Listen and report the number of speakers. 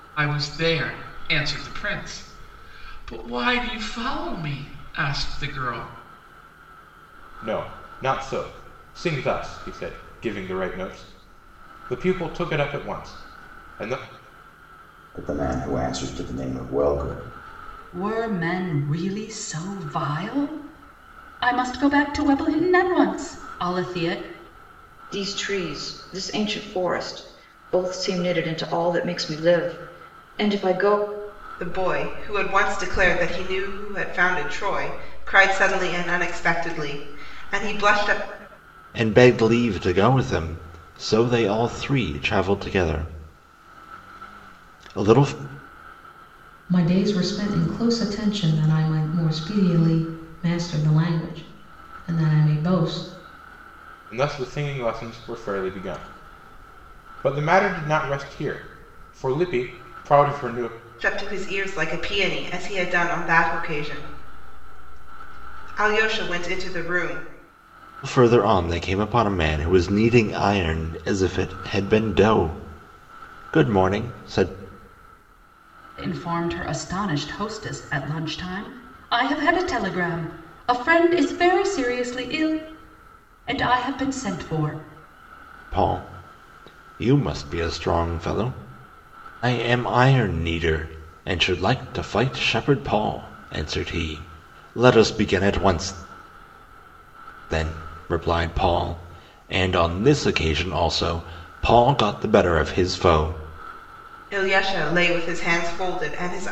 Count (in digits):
8